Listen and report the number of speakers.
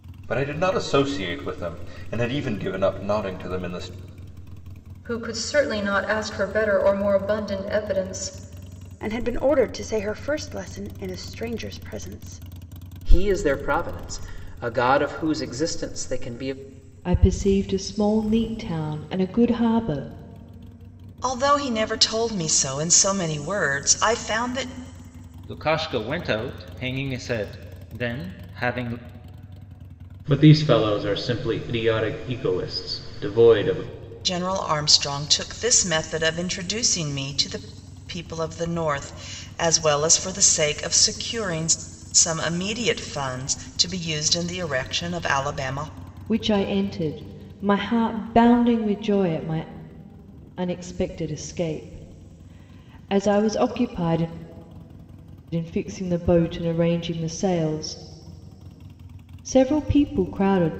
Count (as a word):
eight